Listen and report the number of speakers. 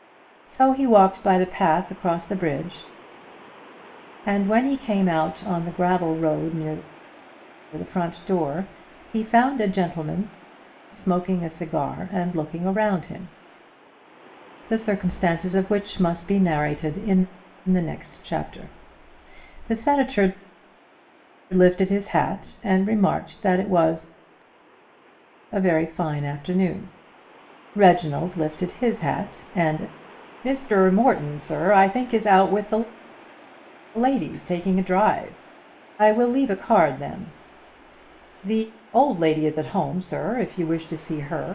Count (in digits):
1